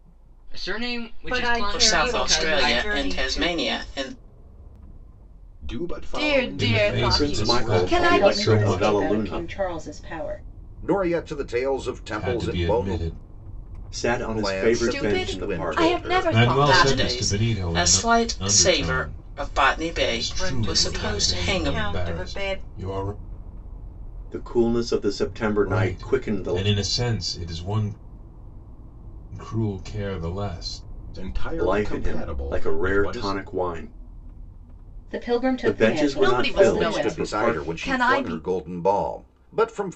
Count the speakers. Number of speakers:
9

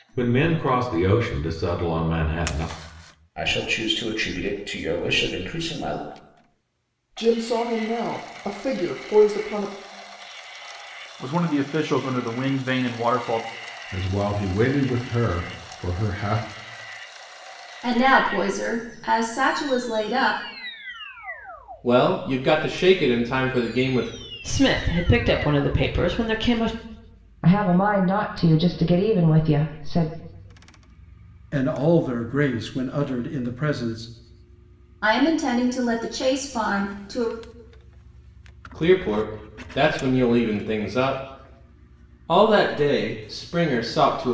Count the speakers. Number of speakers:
10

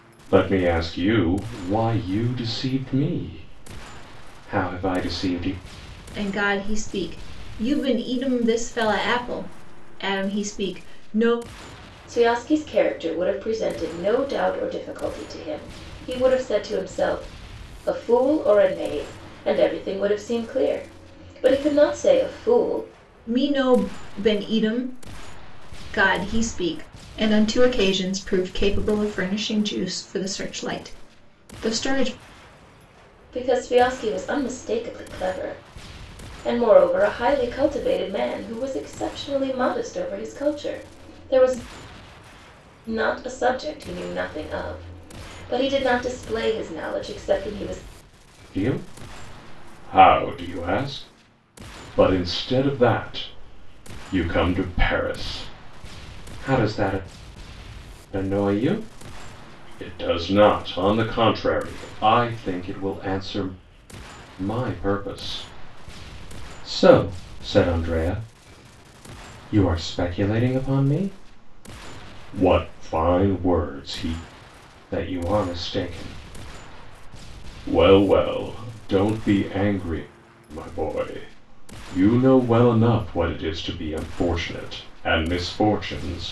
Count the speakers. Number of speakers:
3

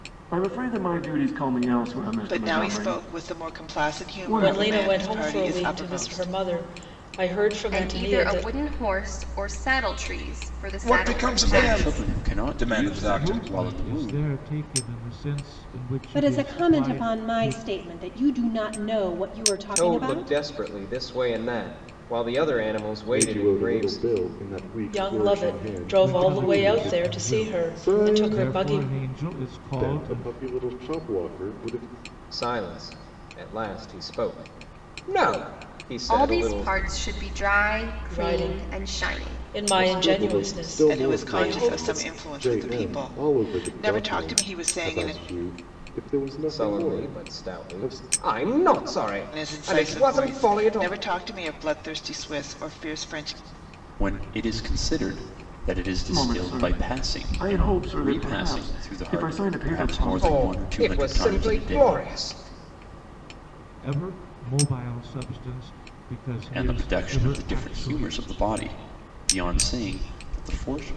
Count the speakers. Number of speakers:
10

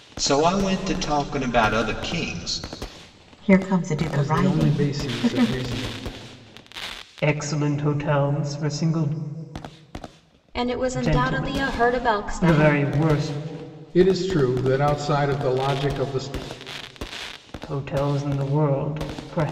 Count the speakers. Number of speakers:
5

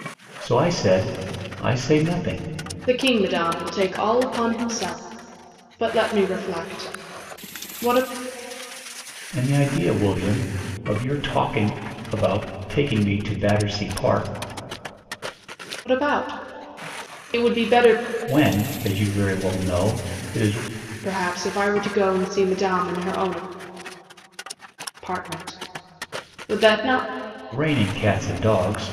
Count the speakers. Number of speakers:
2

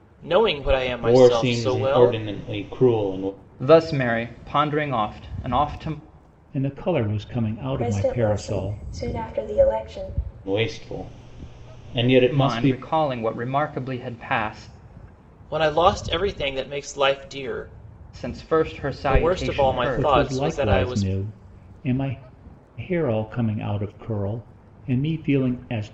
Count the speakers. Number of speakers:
5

